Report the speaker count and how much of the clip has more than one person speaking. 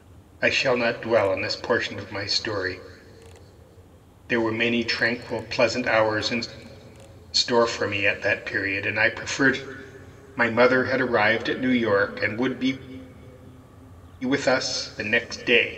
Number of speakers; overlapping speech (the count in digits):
1, no overlap